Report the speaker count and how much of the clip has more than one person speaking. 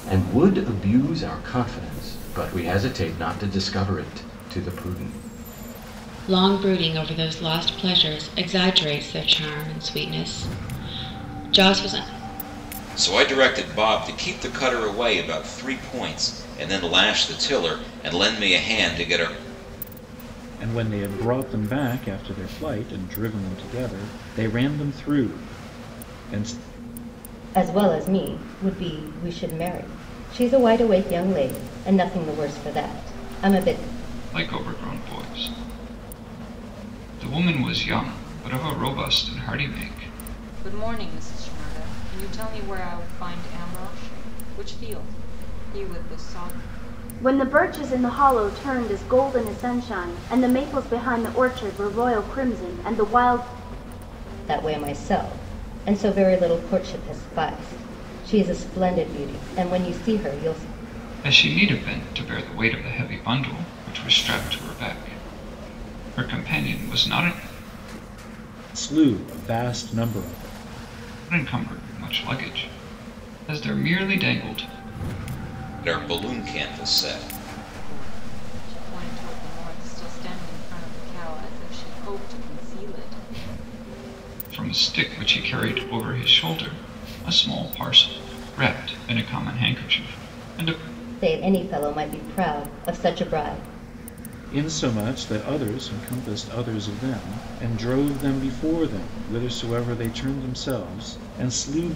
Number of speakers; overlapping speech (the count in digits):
8, no overlap